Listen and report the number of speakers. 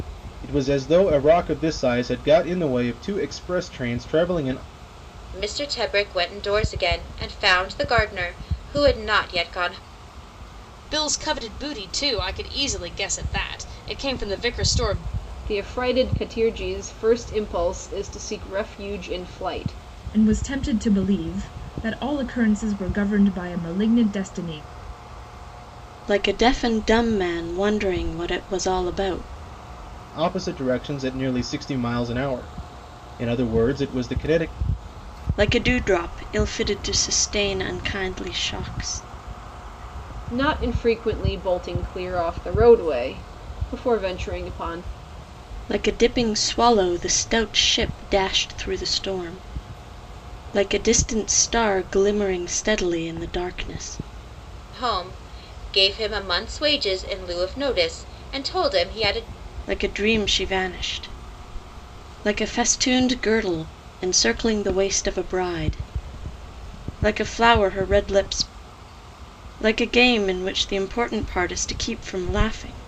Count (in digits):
6